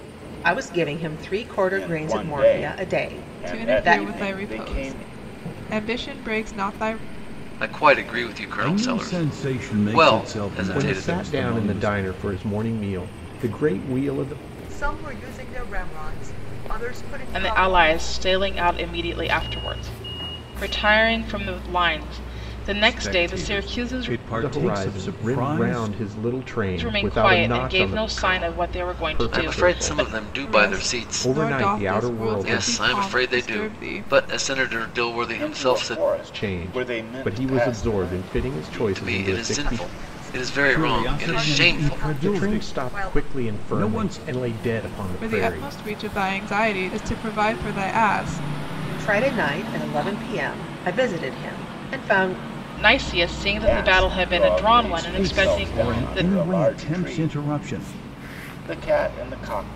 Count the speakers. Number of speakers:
eight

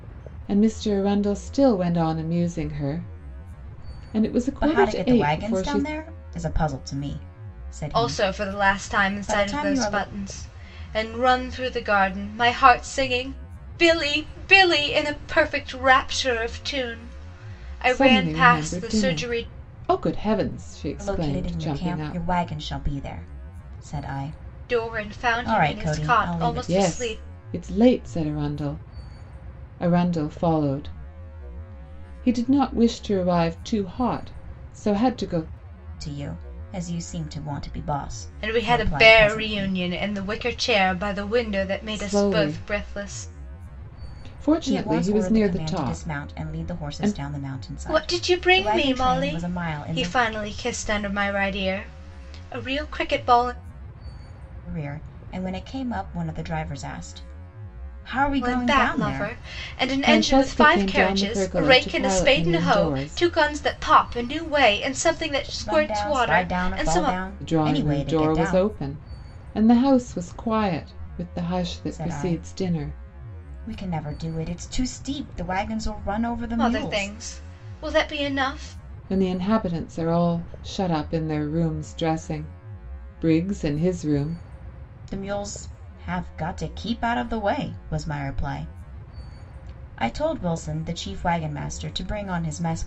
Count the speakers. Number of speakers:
three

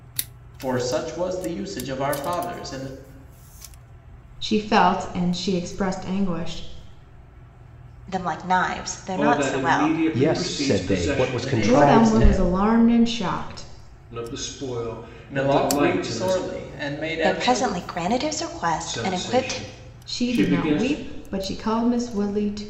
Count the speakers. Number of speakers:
five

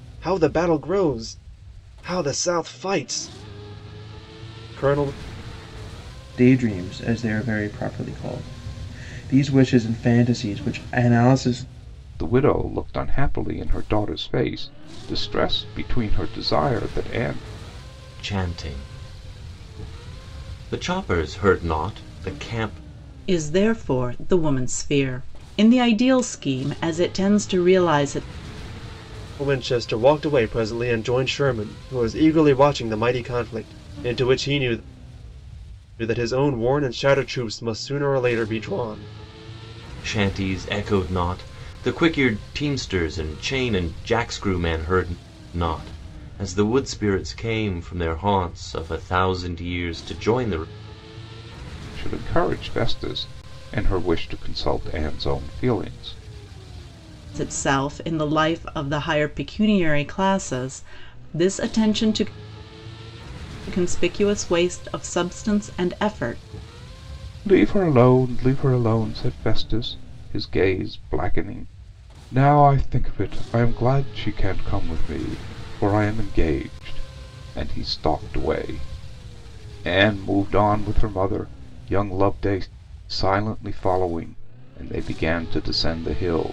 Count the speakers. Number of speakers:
five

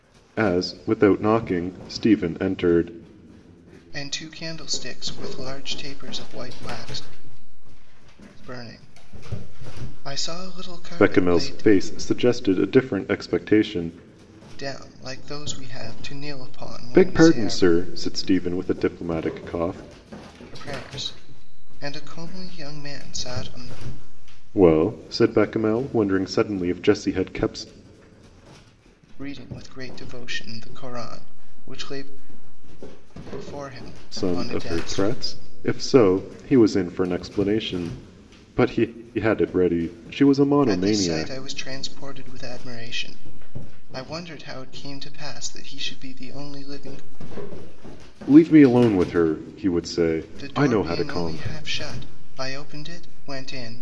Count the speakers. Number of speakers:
two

